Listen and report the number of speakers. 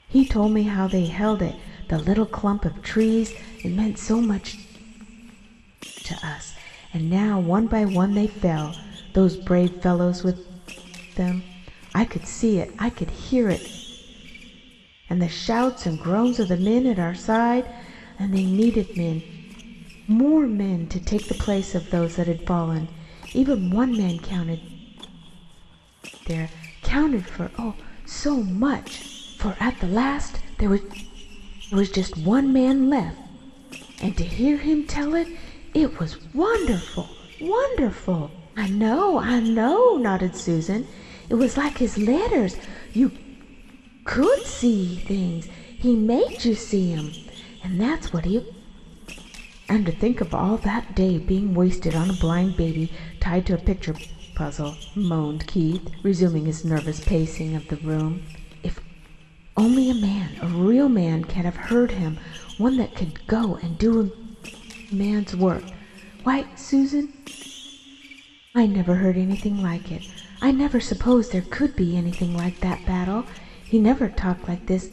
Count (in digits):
1